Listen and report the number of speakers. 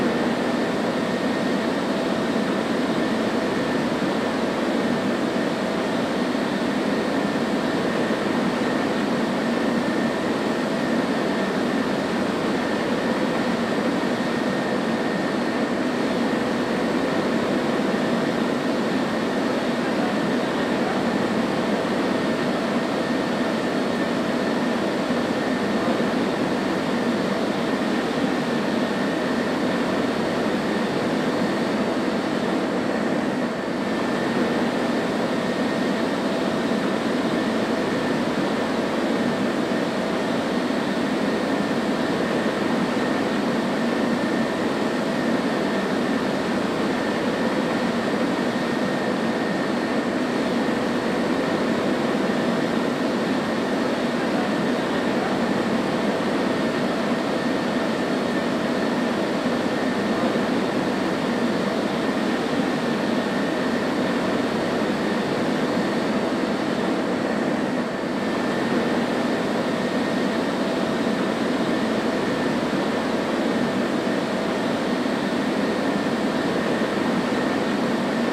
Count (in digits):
0